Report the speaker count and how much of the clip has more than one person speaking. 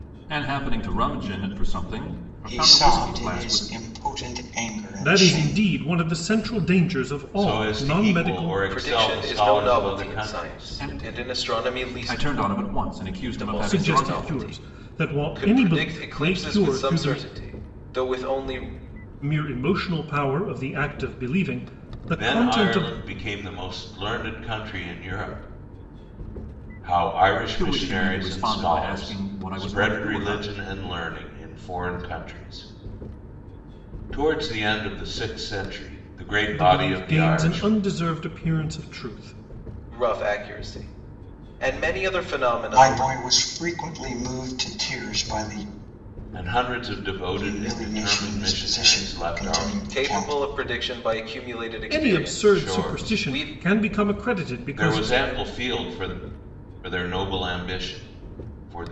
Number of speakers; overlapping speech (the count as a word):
five, about 37%